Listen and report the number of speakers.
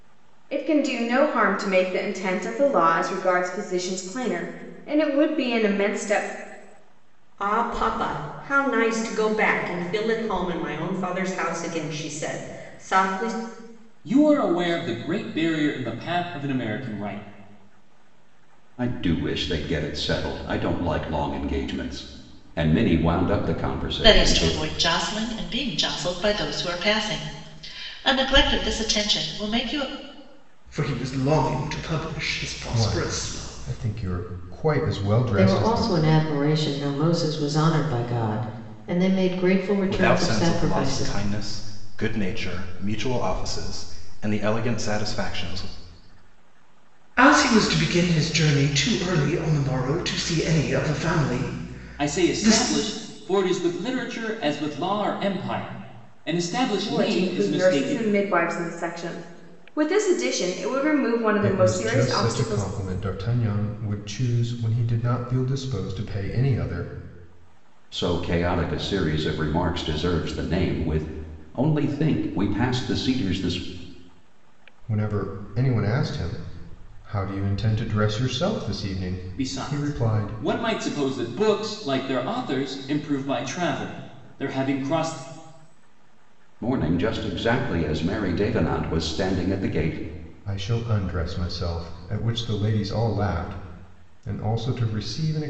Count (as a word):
nine